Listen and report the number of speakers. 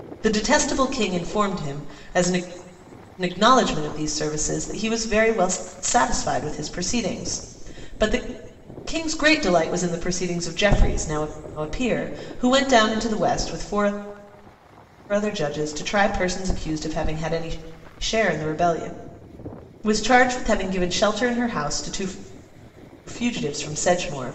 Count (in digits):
1